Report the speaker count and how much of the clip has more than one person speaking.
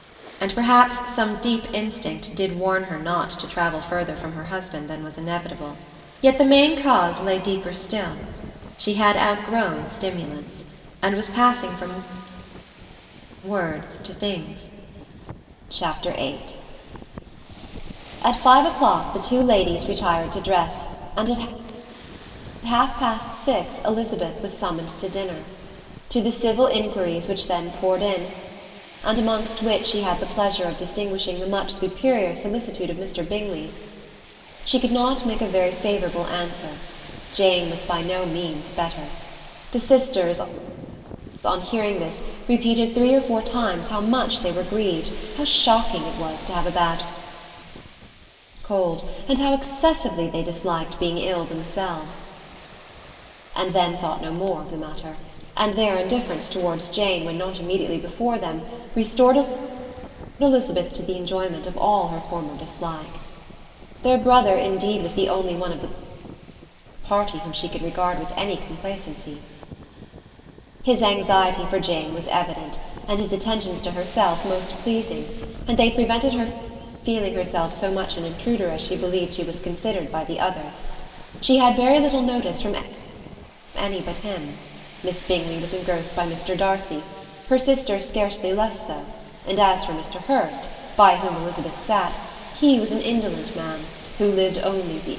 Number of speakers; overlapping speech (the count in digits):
1, no overlap